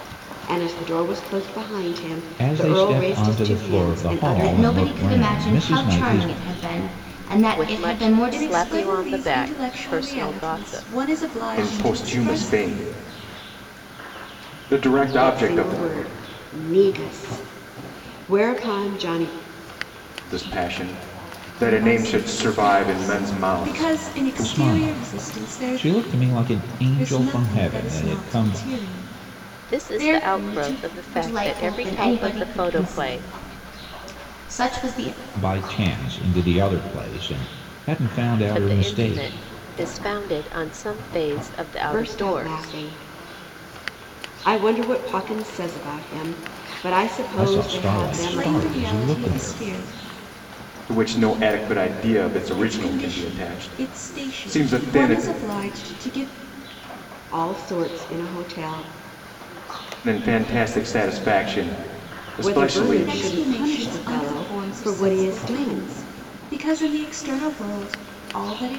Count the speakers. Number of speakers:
6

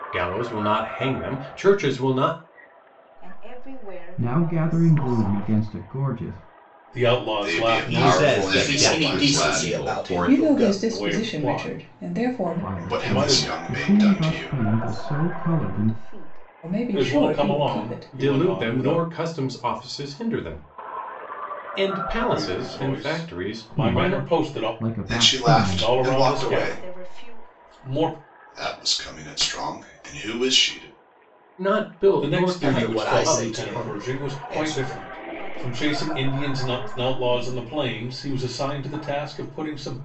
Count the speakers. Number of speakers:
8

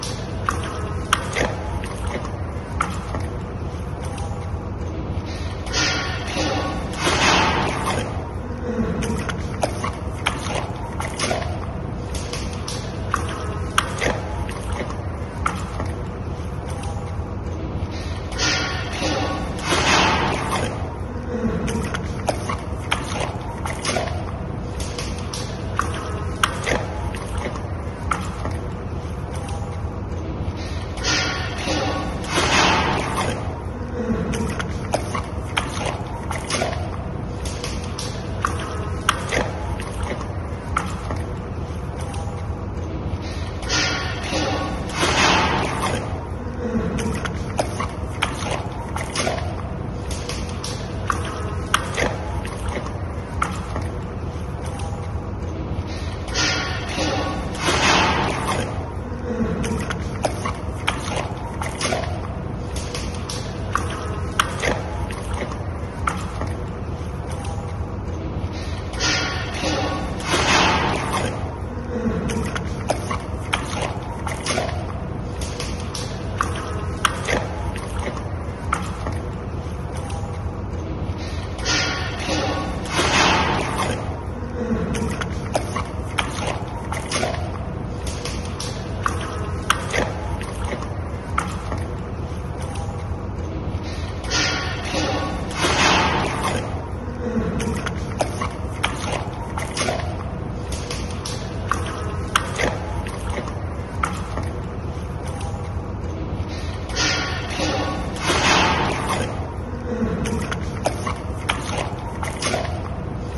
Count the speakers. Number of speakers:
0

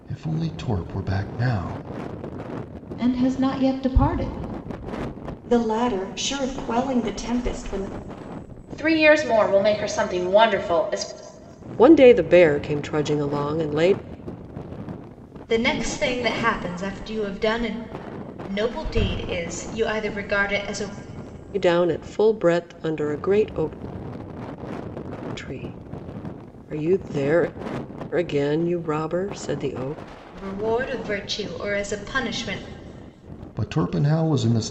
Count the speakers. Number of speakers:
6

